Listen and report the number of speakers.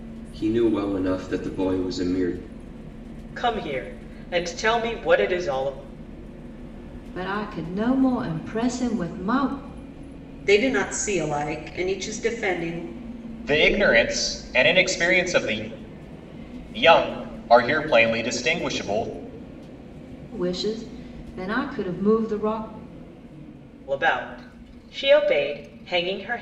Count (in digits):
5